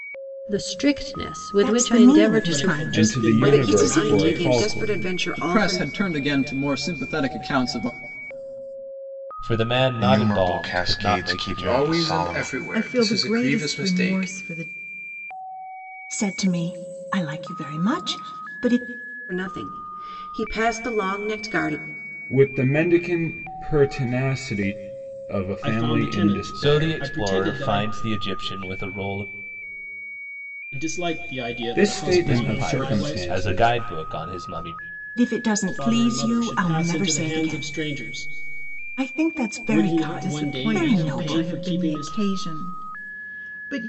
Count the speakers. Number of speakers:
ten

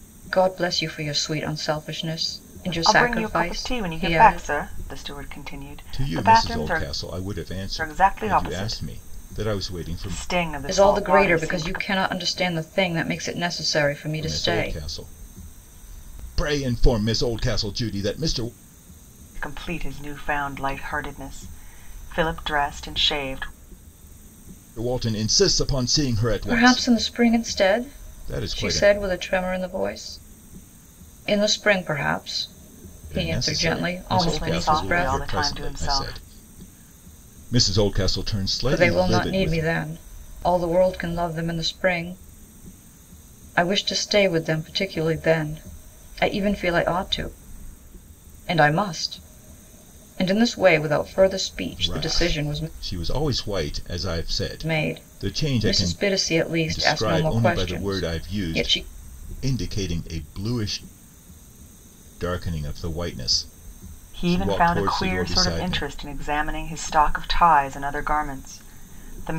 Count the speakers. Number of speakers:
three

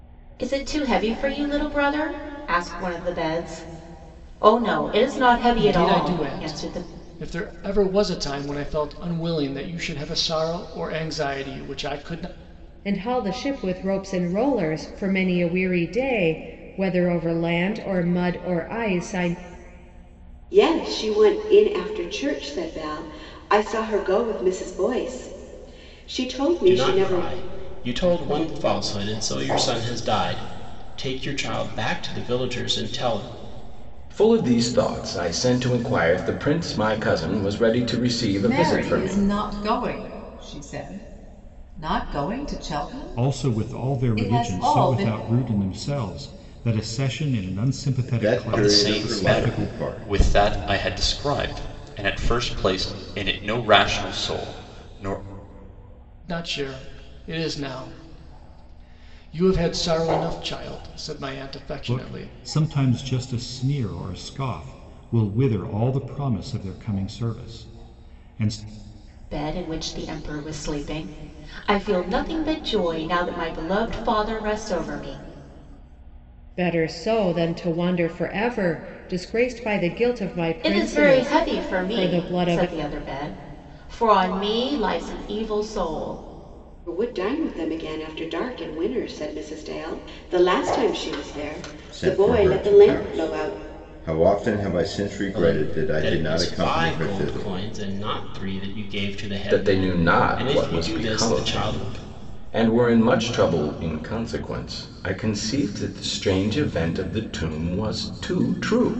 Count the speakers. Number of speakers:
ten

